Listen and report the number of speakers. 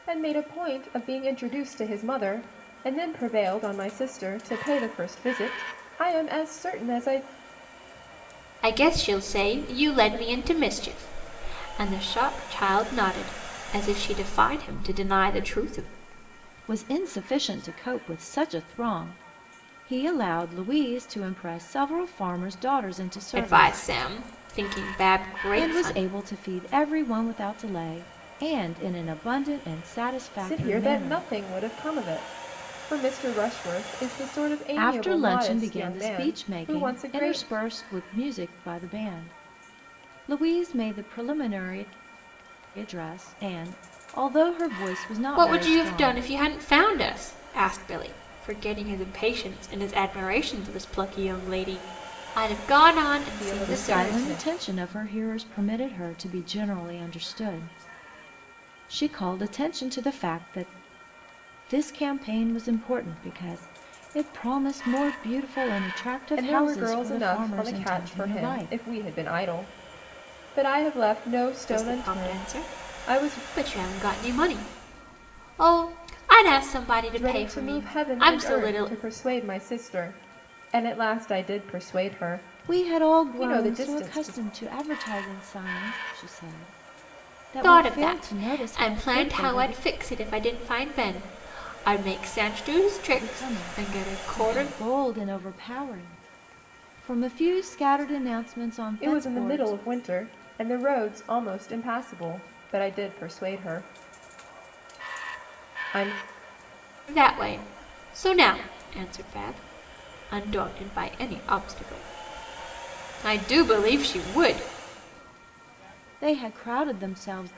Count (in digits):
3